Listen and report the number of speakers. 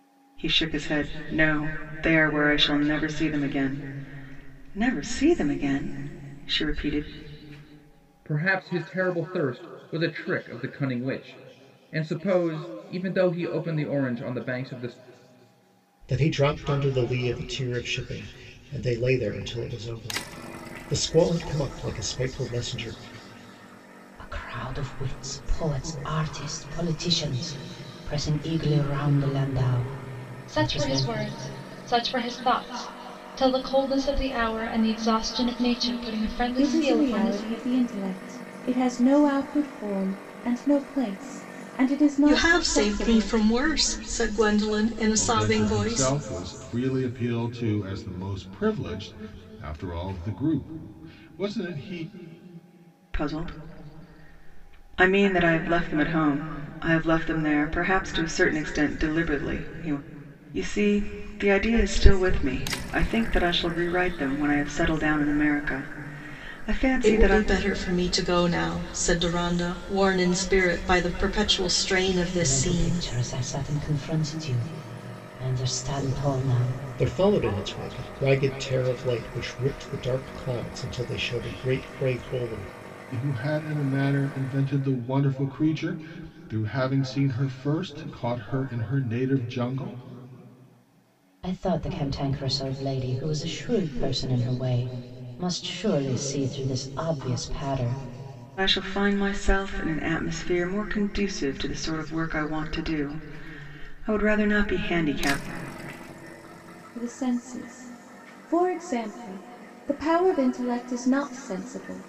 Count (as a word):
eight